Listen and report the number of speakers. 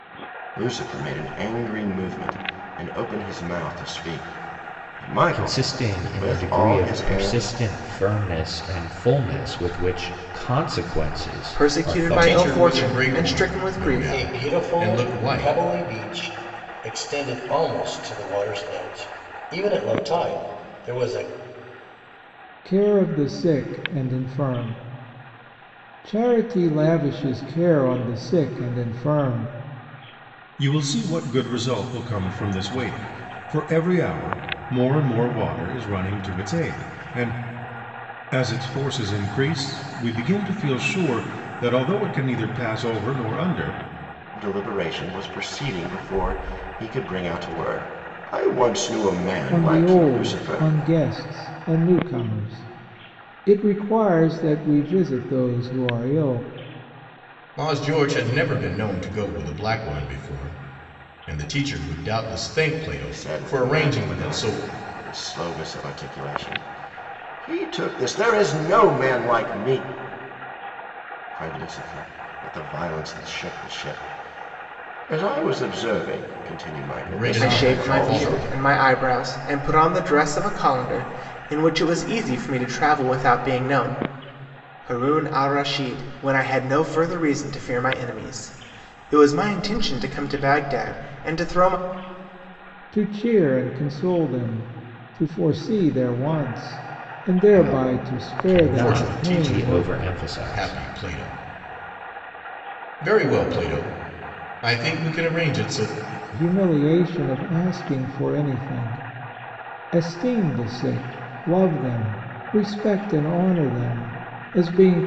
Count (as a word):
seven